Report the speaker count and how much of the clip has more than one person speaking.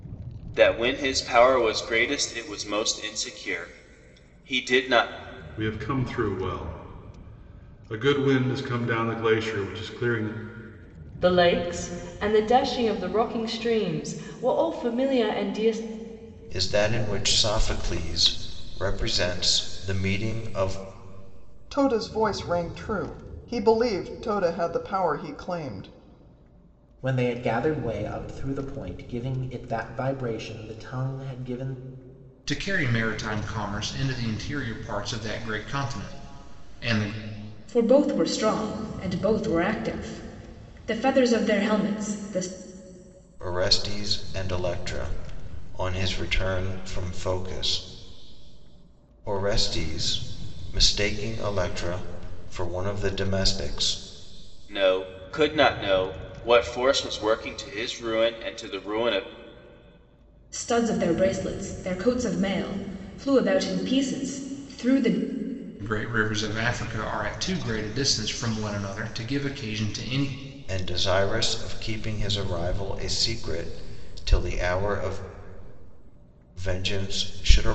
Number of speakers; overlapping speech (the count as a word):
eight, no overlap